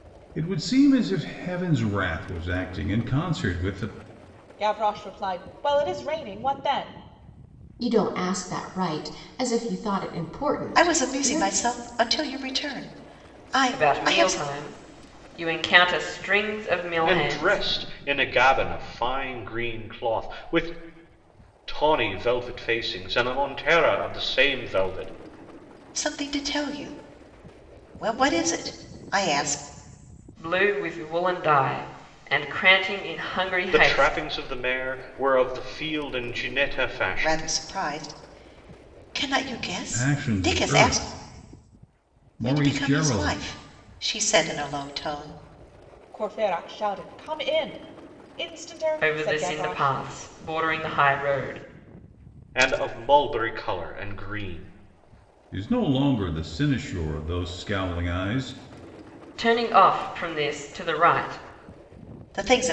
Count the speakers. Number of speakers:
six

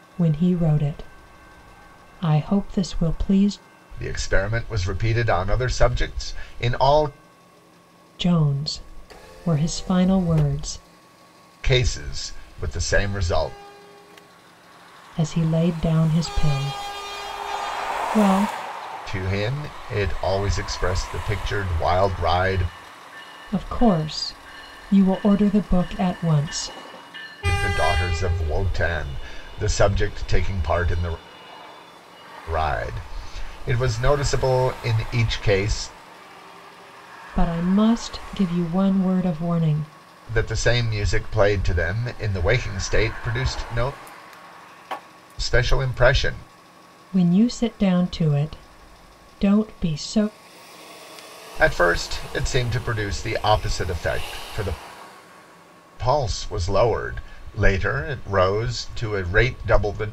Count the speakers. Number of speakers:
two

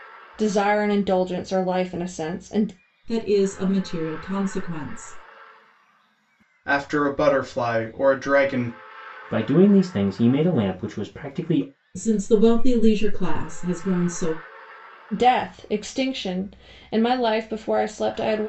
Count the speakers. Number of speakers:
four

